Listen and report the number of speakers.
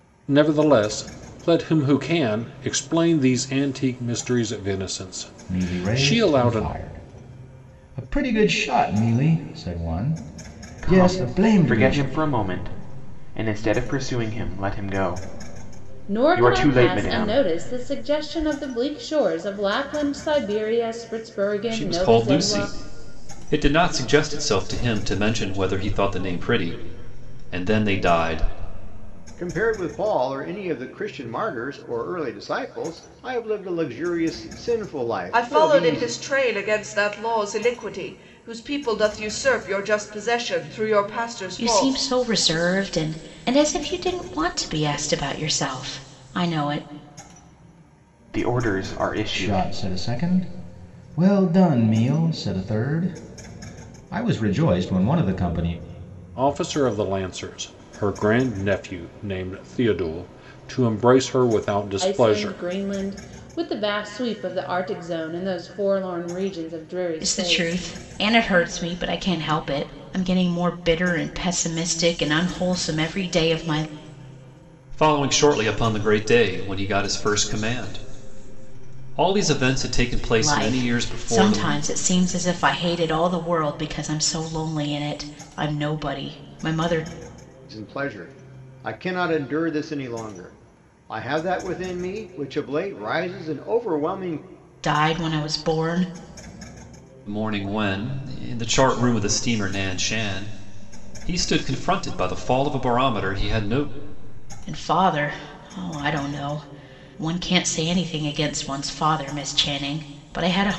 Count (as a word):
eight